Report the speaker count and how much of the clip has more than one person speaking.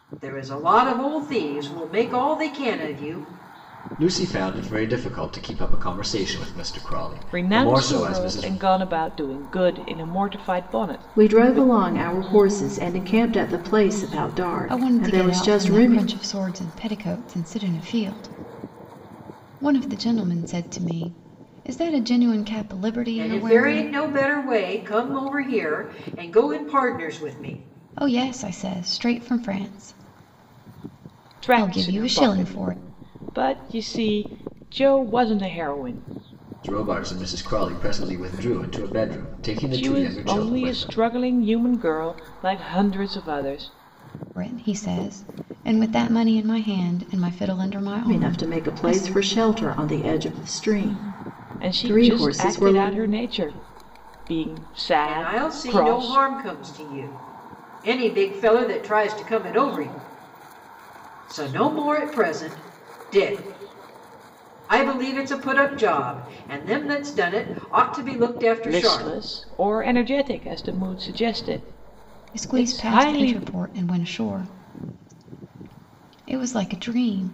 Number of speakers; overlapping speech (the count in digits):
5, about 15%